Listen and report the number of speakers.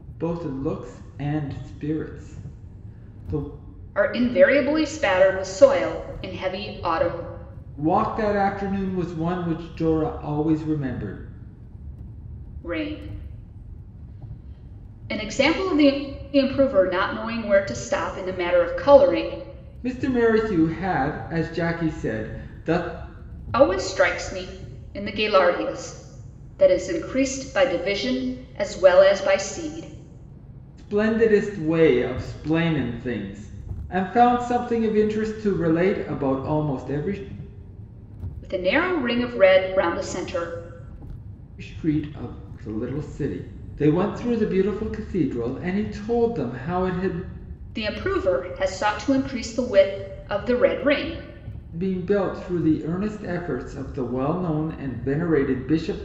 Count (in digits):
2